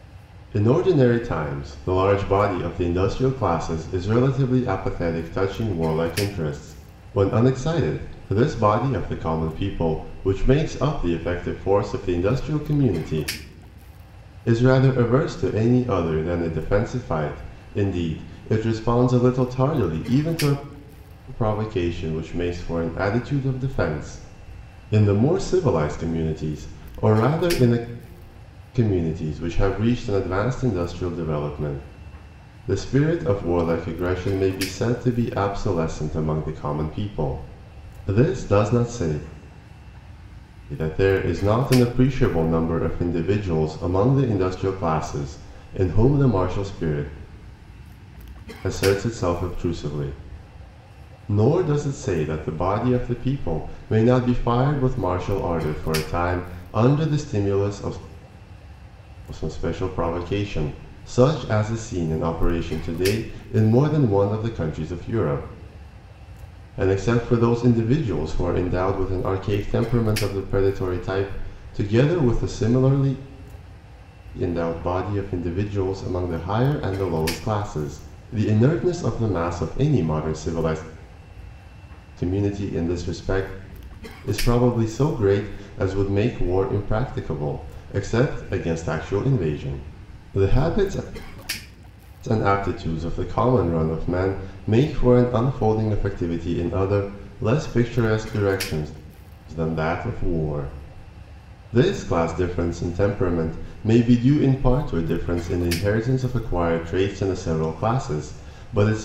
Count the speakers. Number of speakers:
one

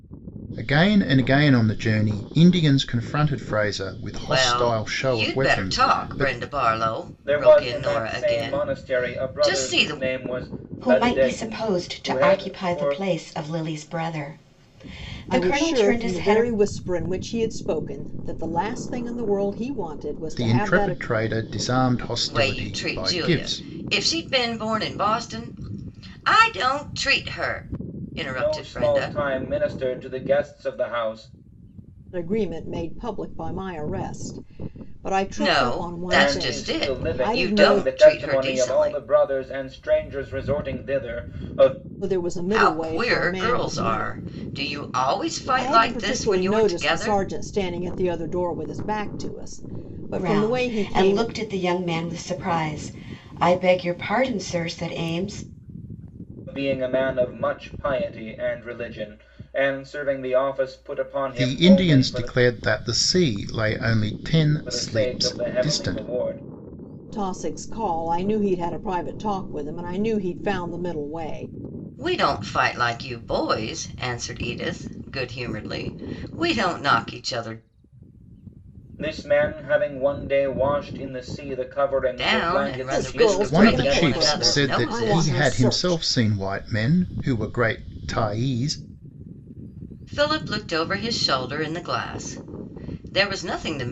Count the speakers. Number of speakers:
five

